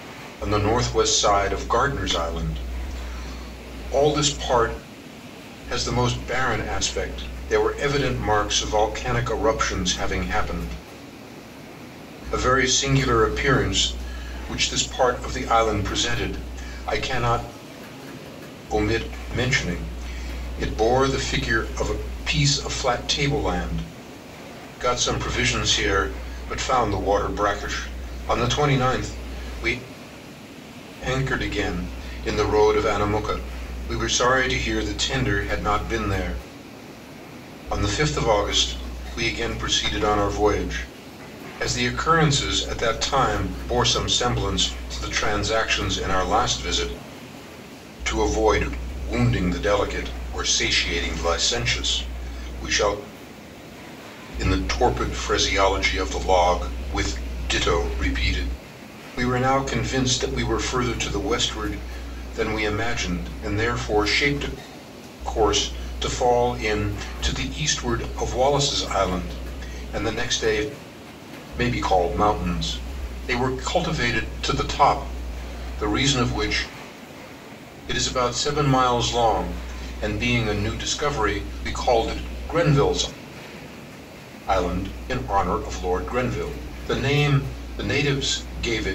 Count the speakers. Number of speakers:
one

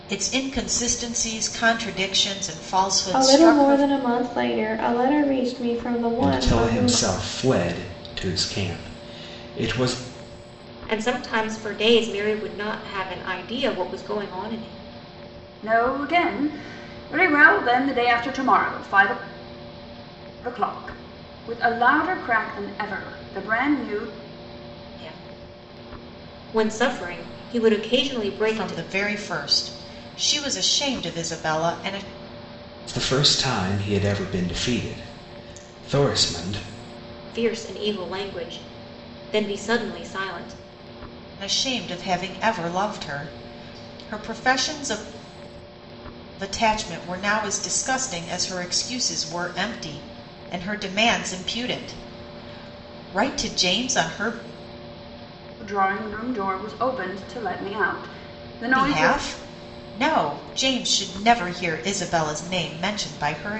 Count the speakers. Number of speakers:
five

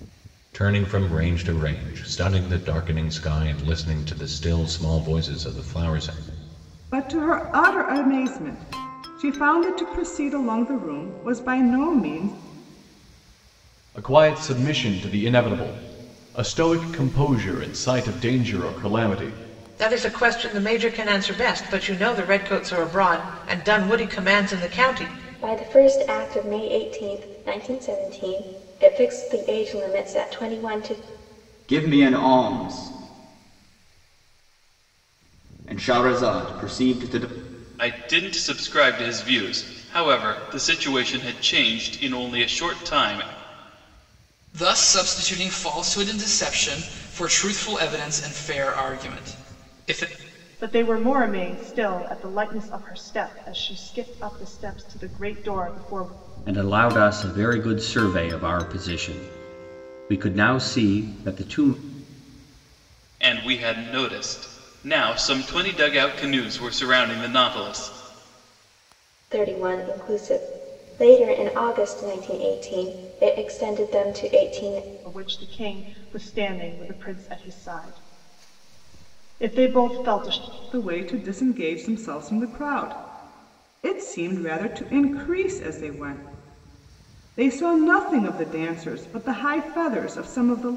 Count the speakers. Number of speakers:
ten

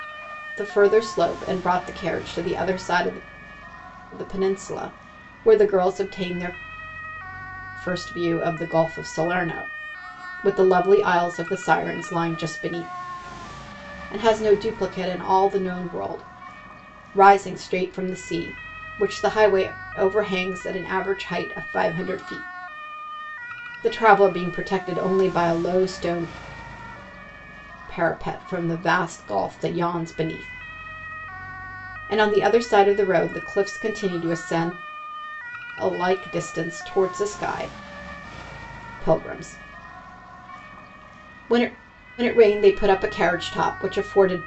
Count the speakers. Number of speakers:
one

